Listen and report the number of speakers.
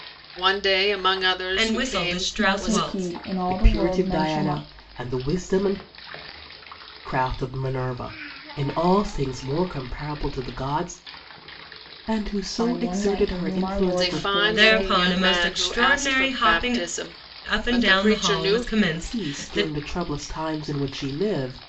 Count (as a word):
four